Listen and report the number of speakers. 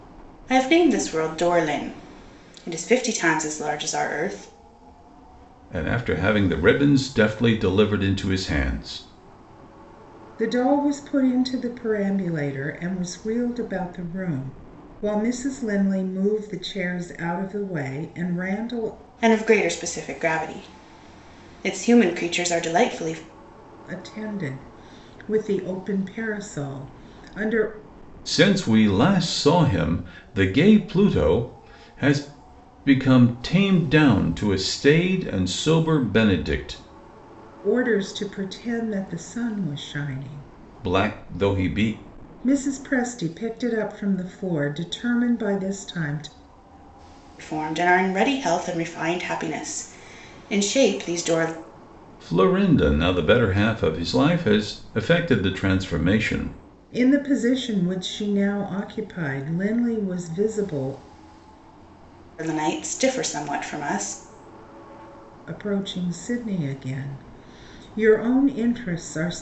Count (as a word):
three